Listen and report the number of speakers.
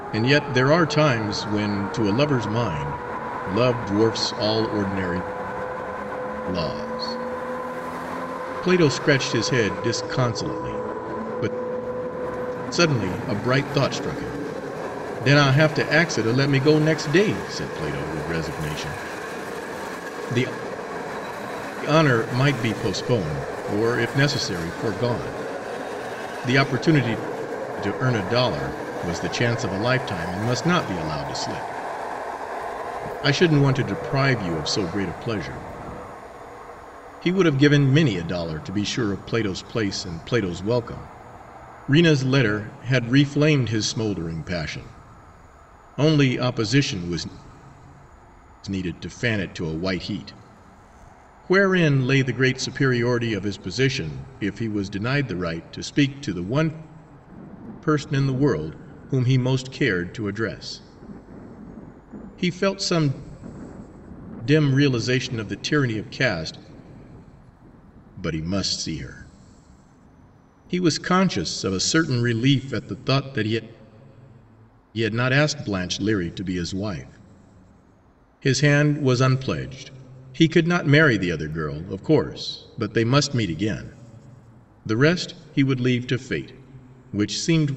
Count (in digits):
1